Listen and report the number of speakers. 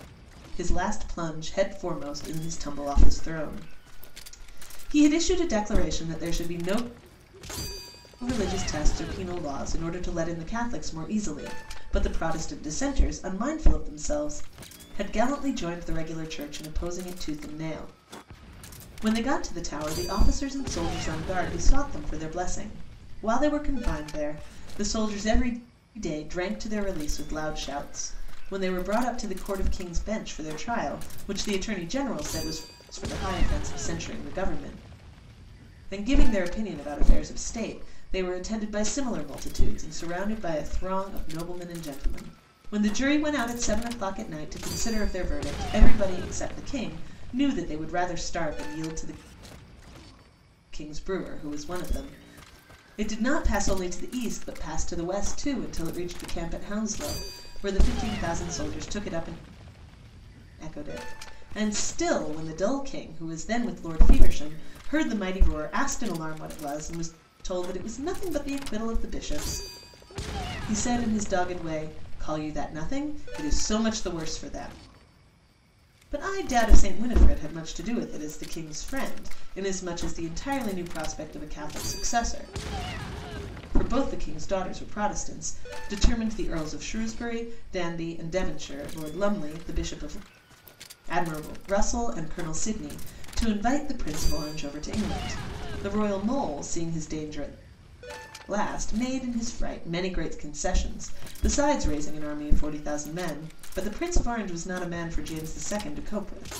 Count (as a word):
one